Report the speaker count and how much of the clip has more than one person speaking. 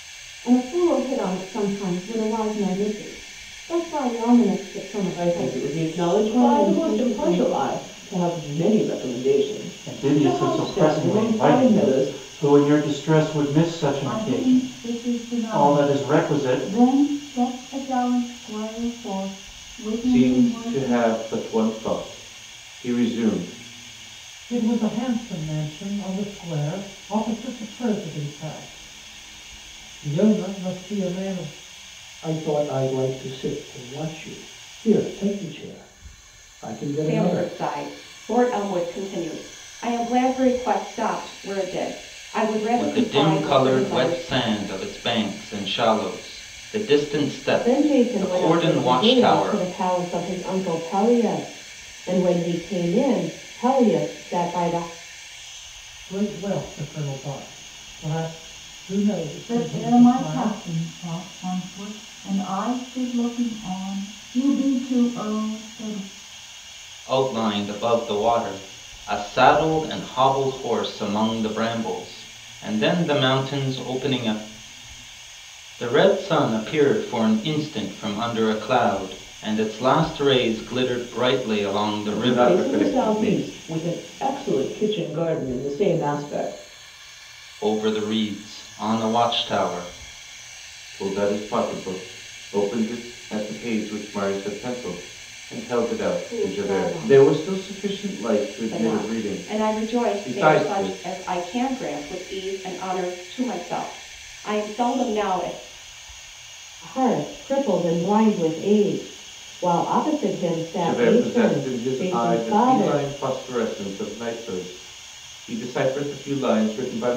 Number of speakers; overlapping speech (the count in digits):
10, about 18%